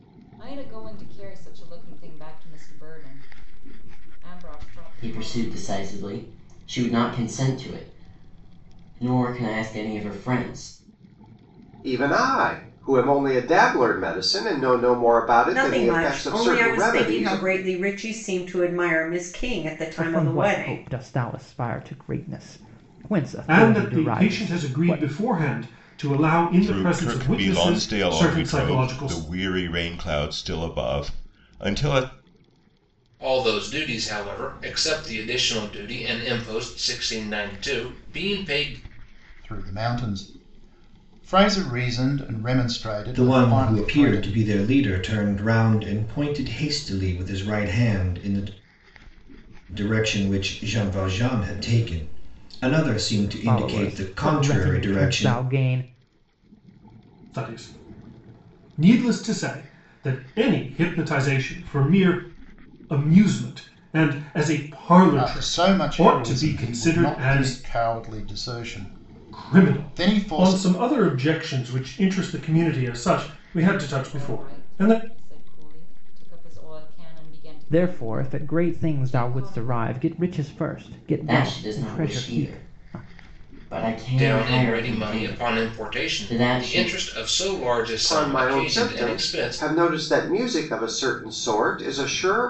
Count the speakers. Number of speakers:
10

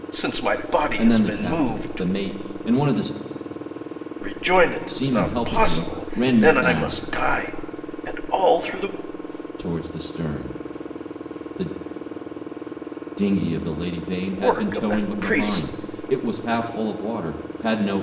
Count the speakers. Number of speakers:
2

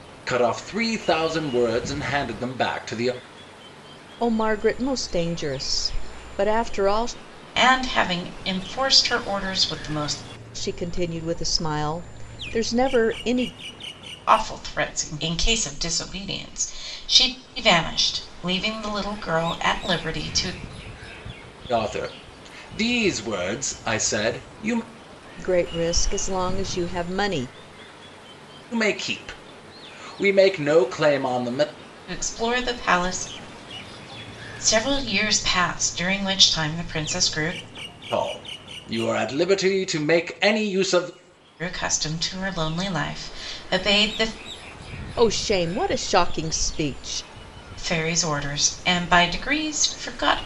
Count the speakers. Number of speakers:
3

